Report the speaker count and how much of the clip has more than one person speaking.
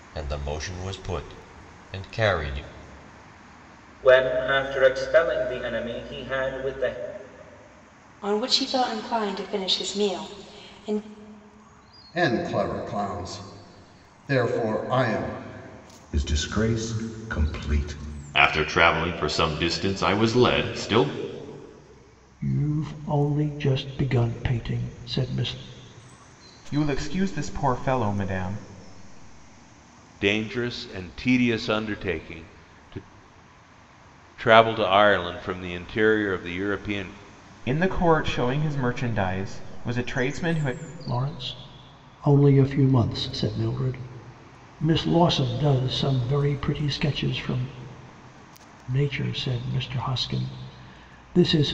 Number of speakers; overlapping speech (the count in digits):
9, no overlap